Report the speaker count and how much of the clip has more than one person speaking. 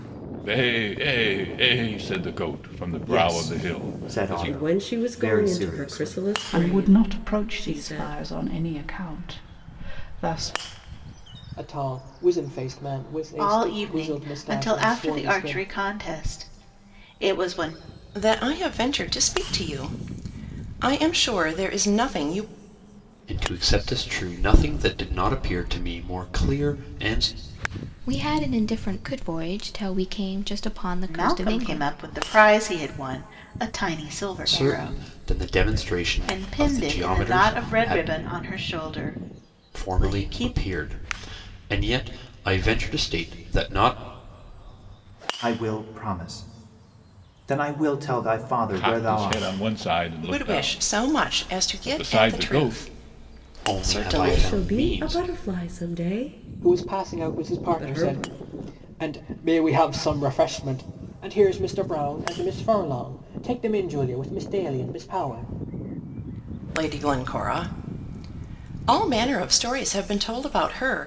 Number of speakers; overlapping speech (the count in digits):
9, about 25%